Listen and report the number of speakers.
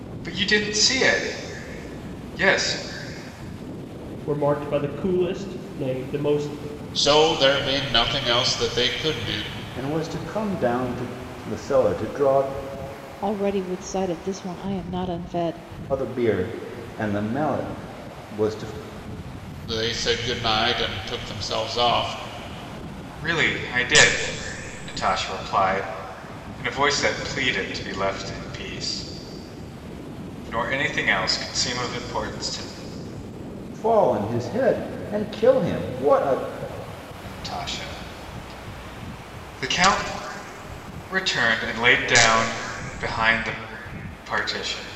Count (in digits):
5